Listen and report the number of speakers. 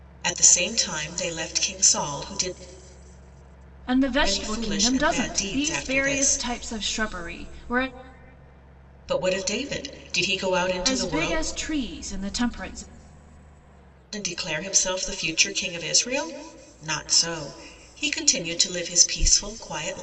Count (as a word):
two